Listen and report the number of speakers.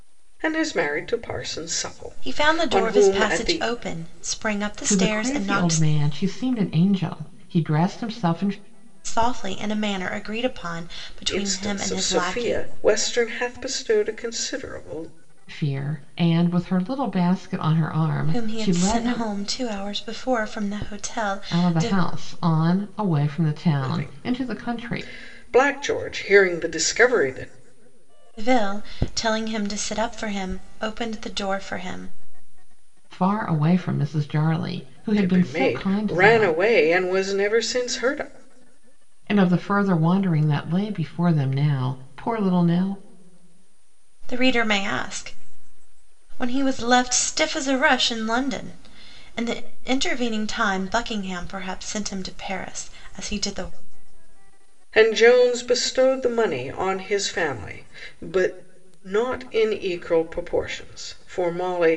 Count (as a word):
three